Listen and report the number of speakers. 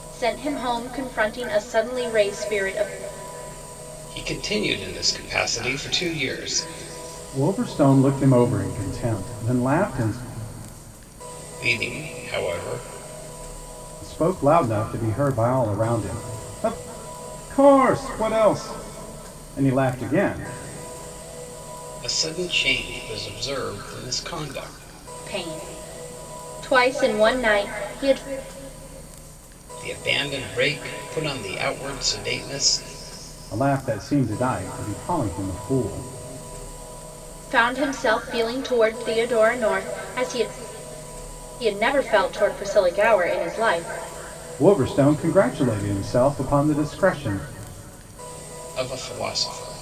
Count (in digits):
3